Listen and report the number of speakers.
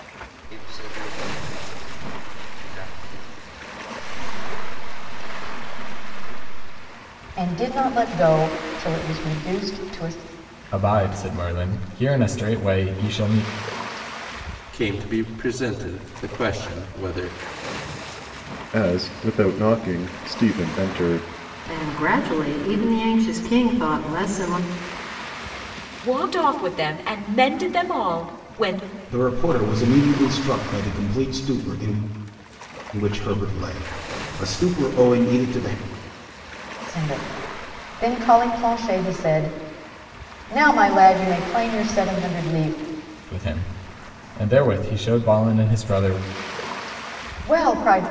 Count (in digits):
9